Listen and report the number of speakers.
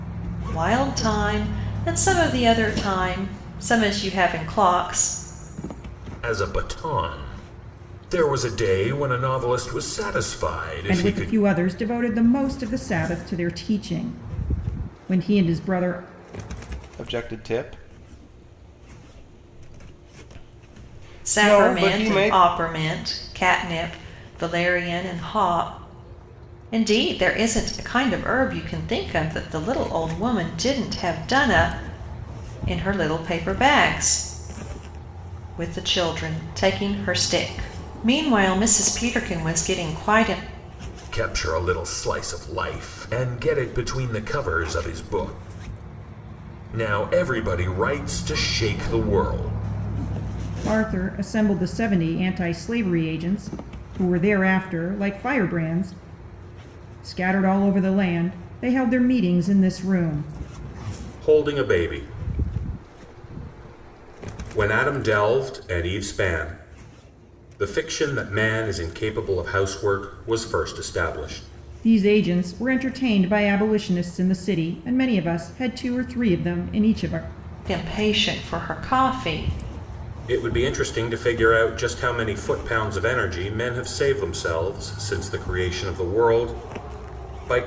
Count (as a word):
four